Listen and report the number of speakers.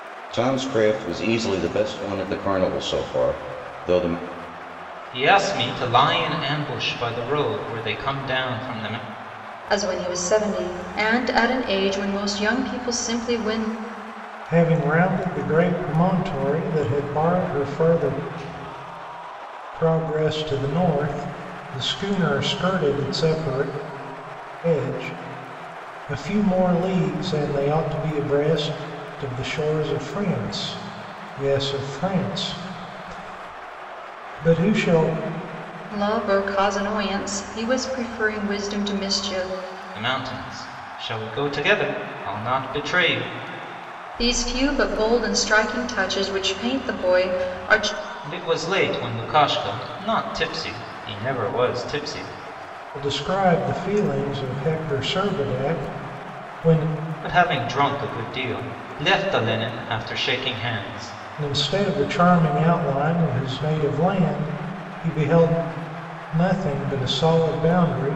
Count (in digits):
4